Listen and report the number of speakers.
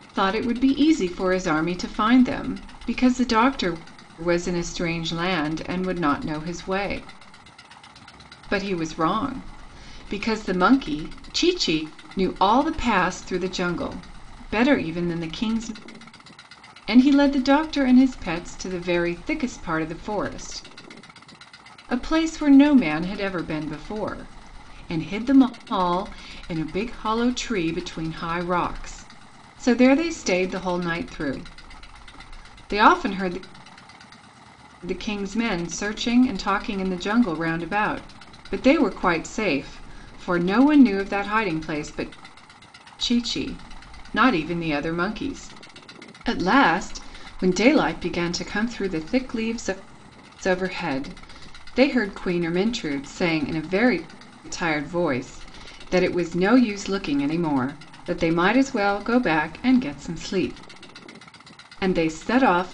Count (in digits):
1